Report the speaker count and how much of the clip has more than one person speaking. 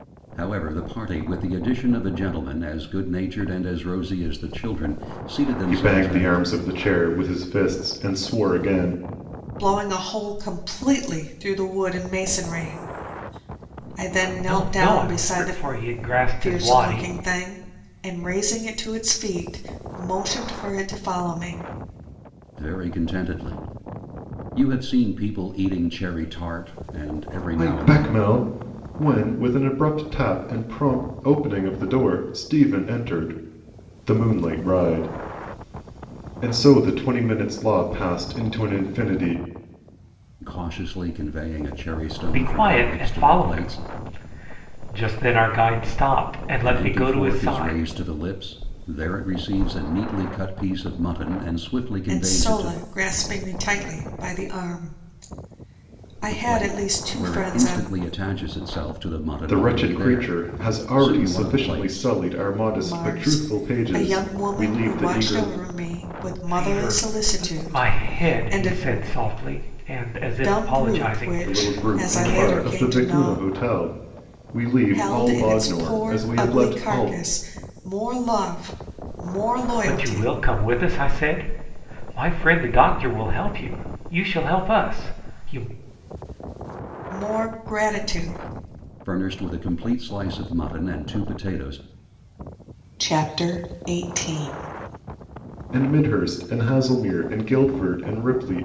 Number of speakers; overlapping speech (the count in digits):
4, about 22%